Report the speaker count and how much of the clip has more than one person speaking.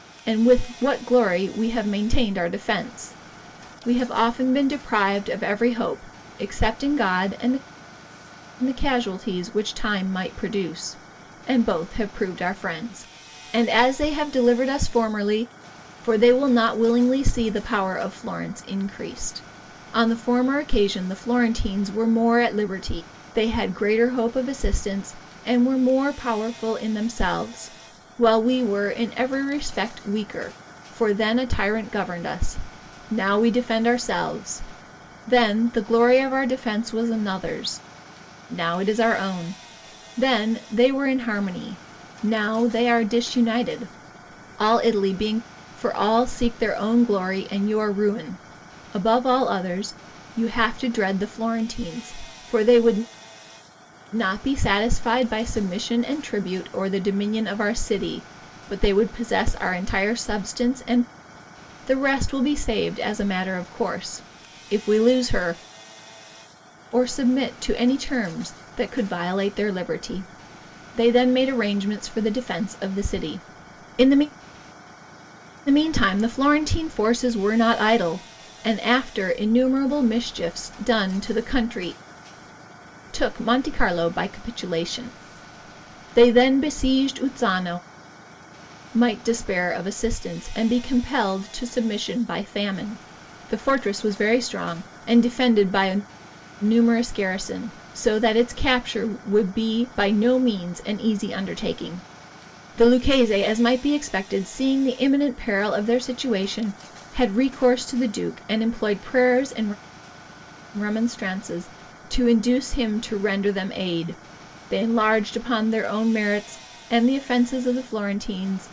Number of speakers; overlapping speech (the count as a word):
one, no overlap